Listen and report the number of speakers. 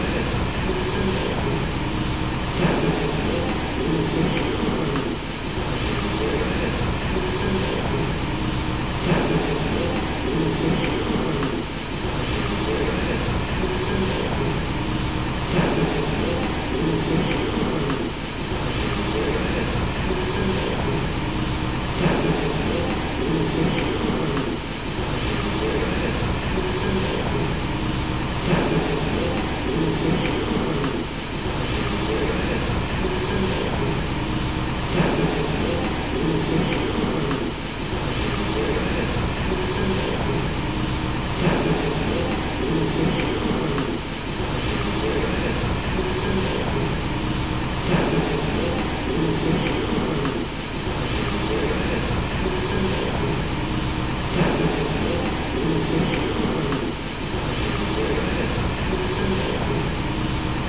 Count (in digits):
0